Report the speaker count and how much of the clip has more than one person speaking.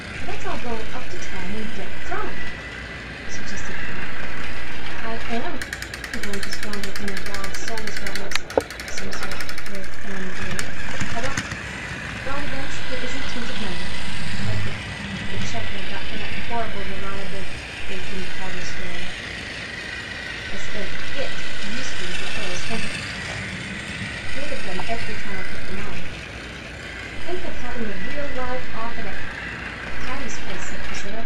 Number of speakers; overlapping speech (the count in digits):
1, no overlap